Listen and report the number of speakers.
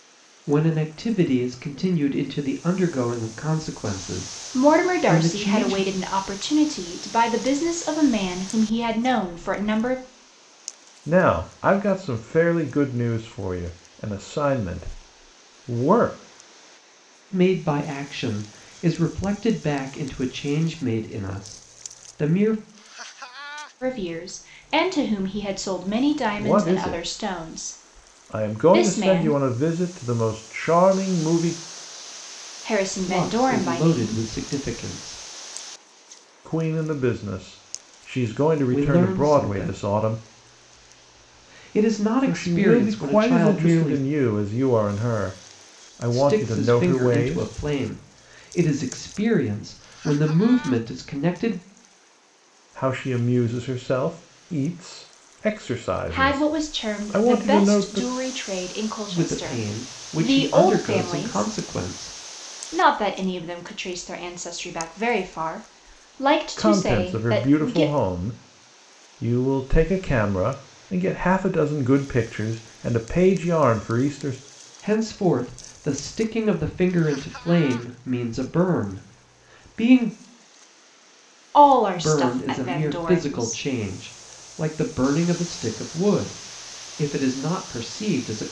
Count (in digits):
3